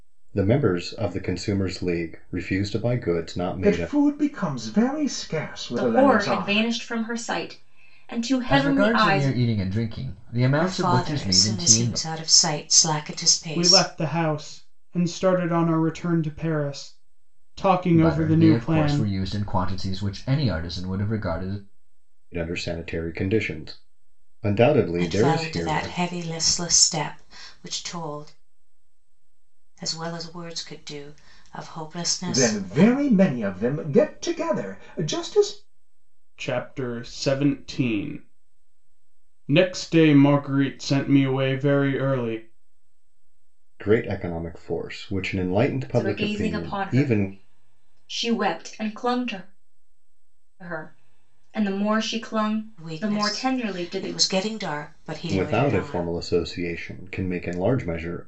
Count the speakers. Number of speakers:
six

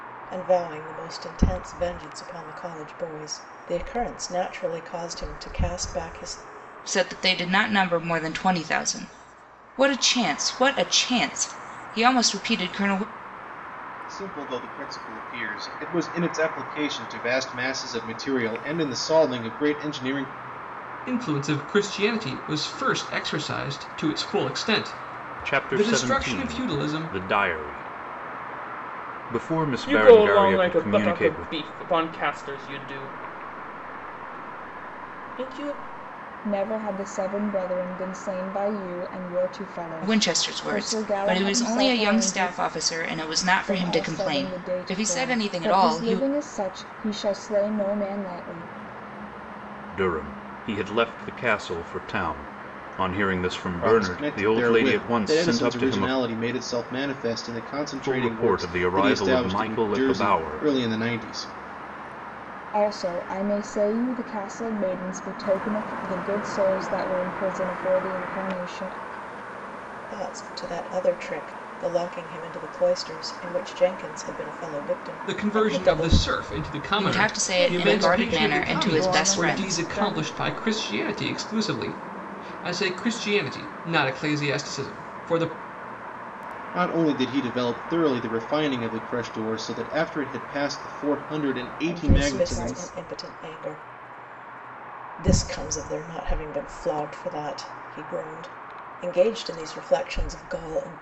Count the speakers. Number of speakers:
seven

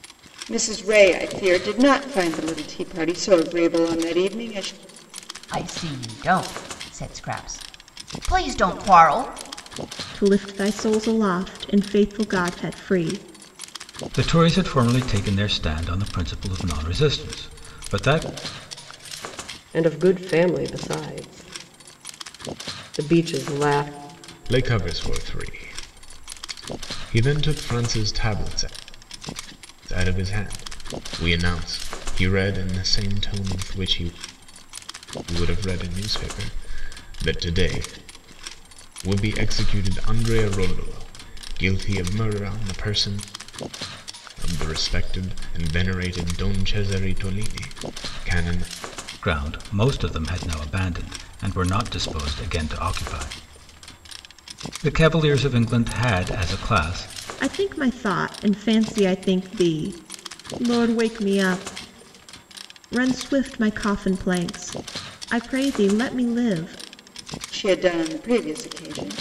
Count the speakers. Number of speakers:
six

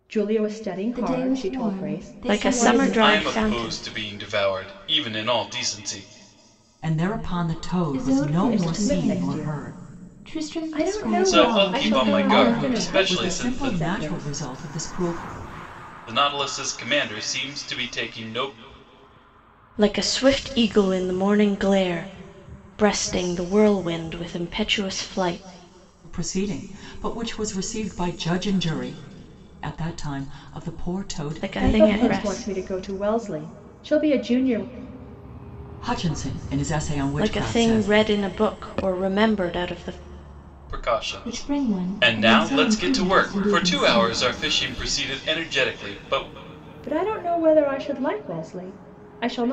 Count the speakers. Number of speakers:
five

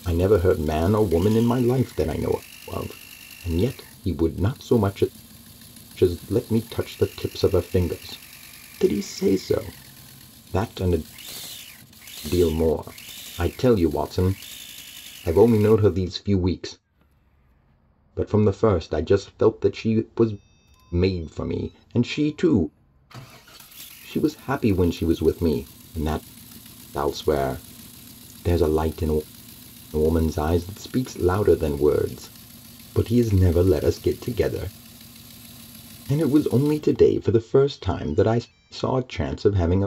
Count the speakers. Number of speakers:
one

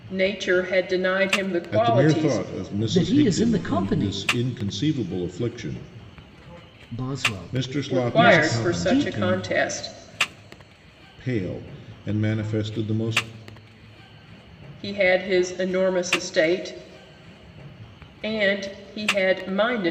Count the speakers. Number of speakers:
three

